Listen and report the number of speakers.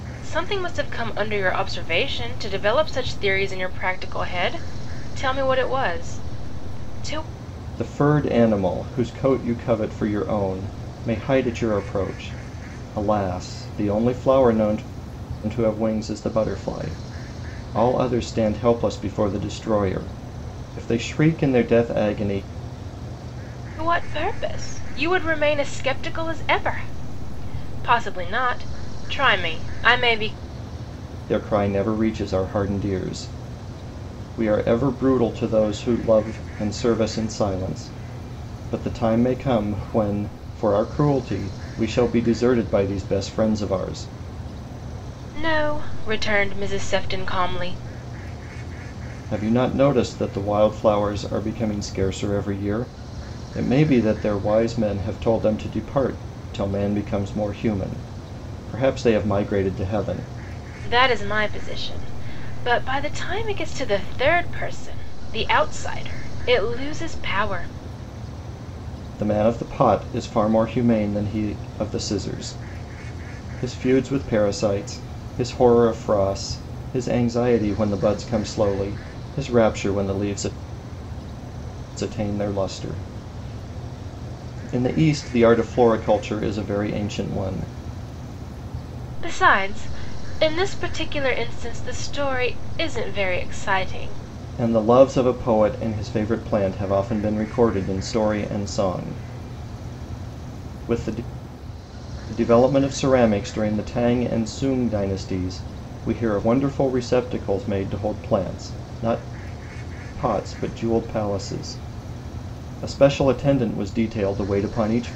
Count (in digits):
2